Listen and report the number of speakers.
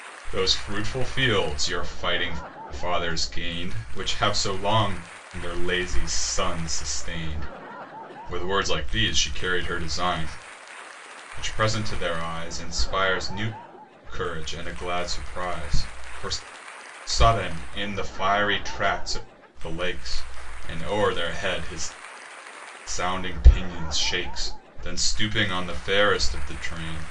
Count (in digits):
1